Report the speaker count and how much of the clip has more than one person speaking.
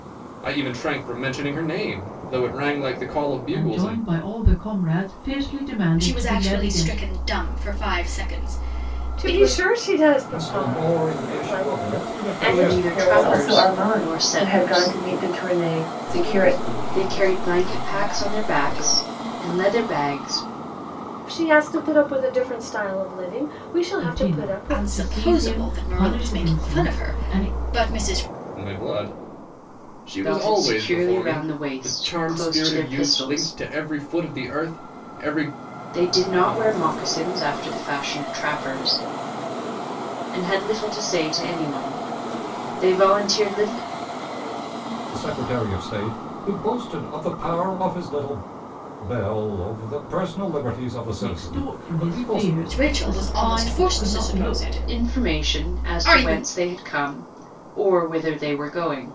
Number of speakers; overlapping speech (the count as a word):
eight, about 36%